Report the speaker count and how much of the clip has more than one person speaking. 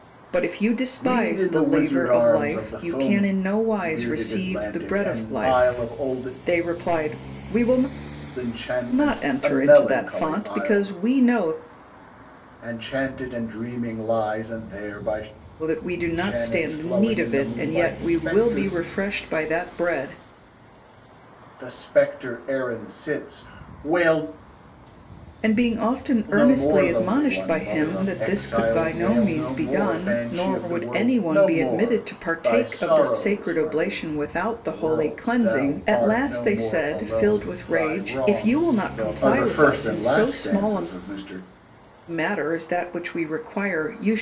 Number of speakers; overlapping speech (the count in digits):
2, about 53%